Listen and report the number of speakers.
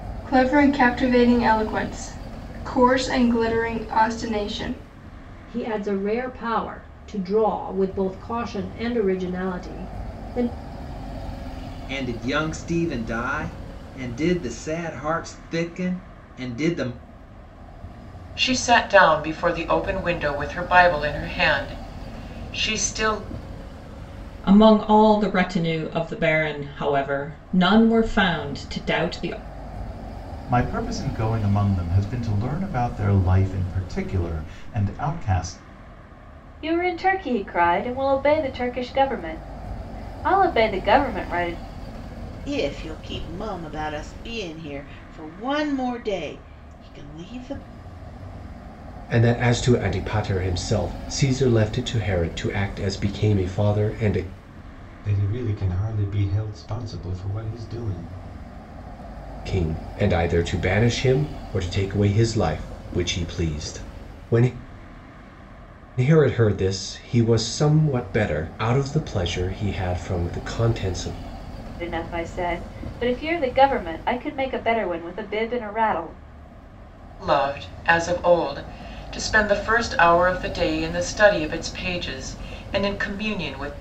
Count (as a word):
ten